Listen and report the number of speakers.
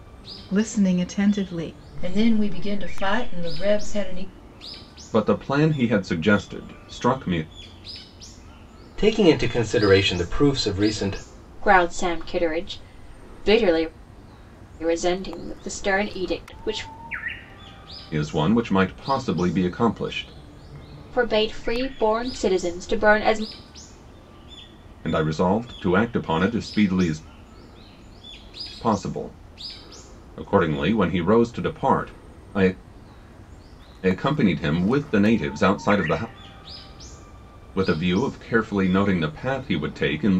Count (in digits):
5